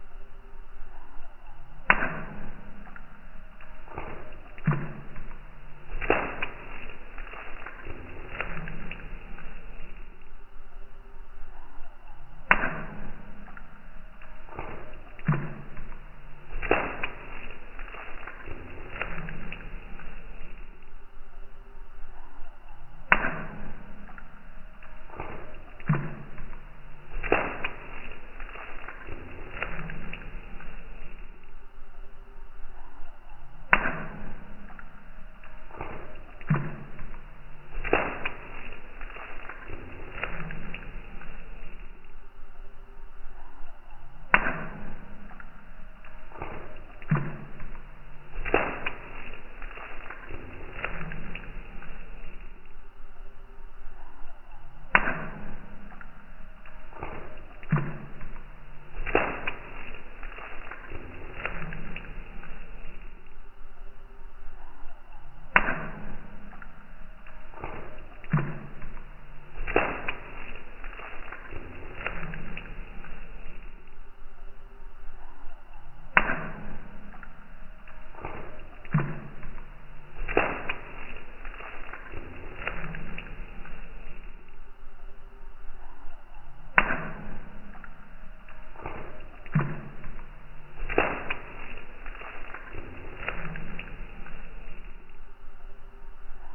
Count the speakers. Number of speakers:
zero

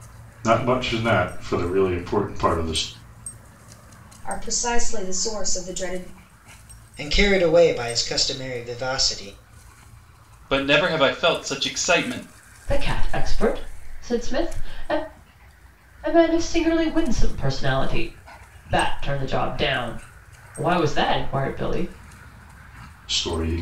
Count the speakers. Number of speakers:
five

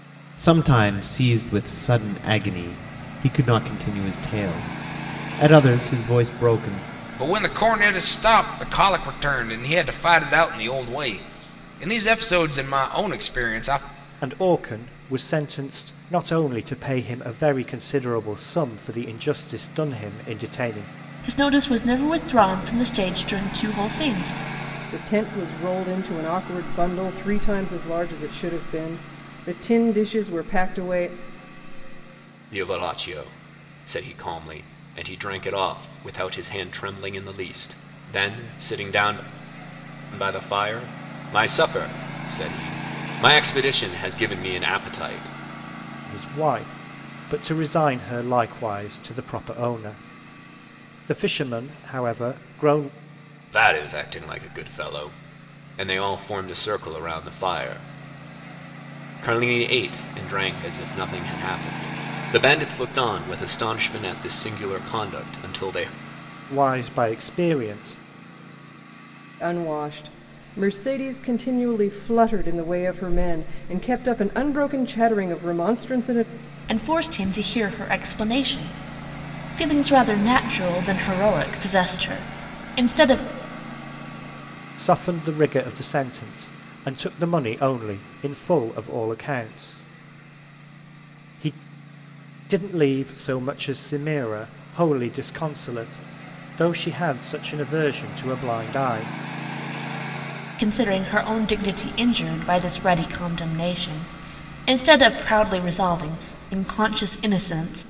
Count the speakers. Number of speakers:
six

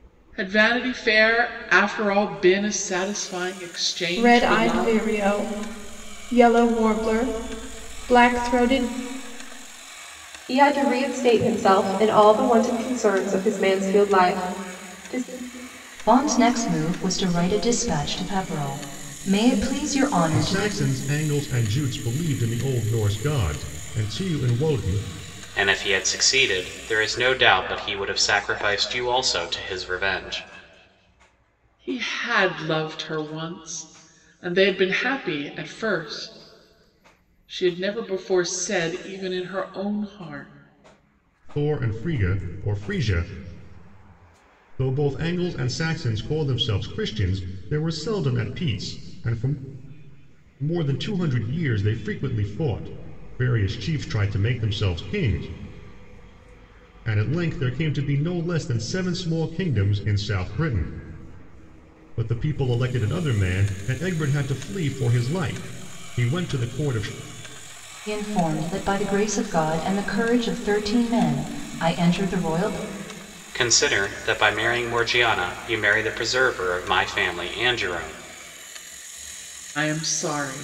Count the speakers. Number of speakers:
six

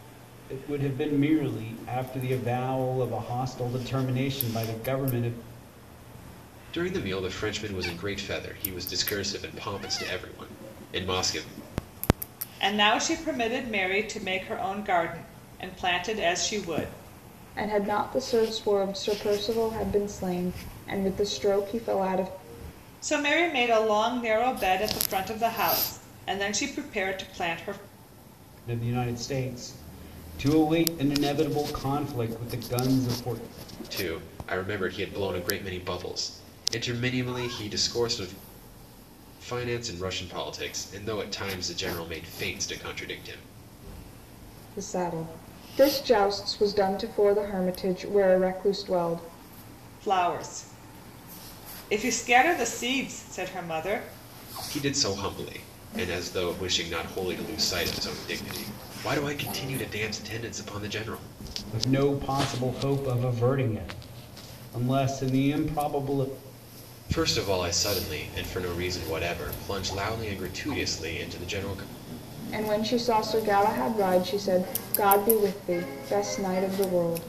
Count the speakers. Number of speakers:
four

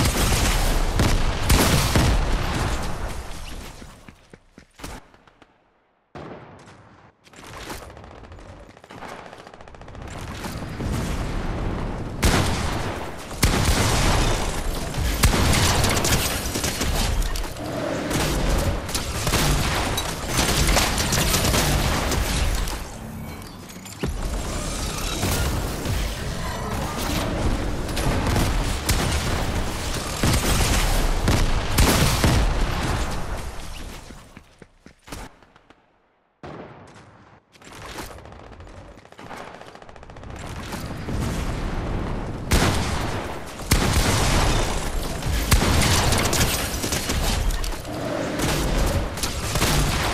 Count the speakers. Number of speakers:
zero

